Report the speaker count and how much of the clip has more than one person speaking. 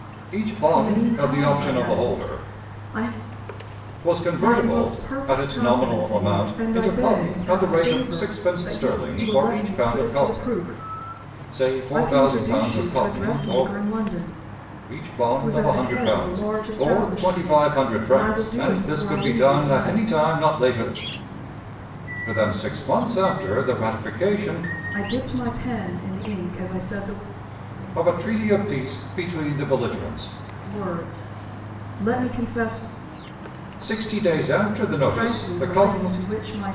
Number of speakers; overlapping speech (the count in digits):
2, about 41%